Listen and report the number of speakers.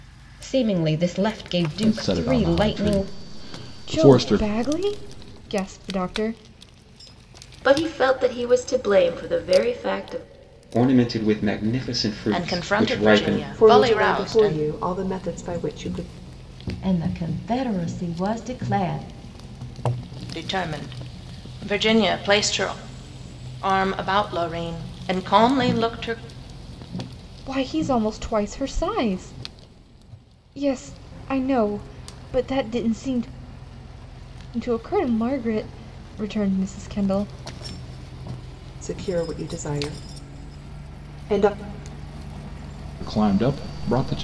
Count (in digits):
8